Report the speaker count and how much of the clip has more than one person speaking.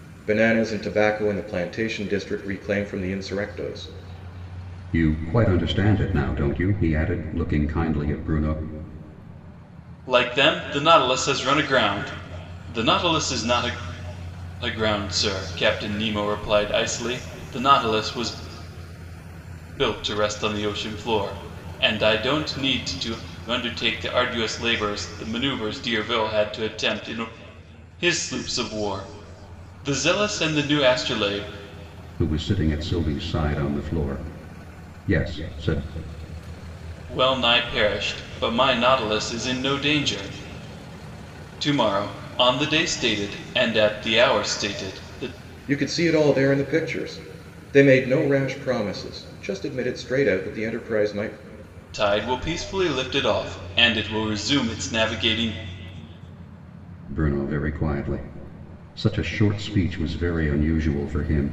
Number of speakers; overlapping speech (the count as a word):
three, no overlap